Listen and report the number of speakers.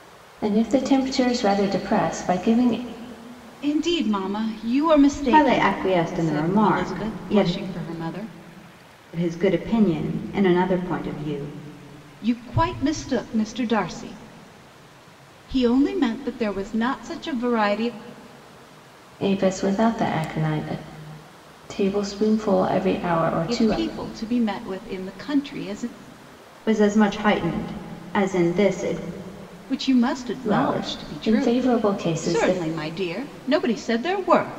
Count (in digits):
3